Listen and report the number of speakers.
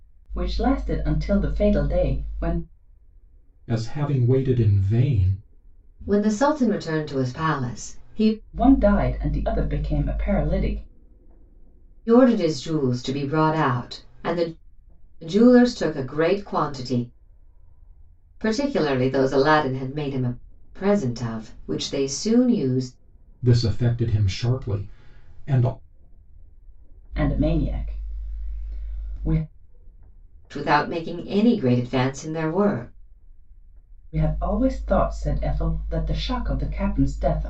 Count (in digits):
3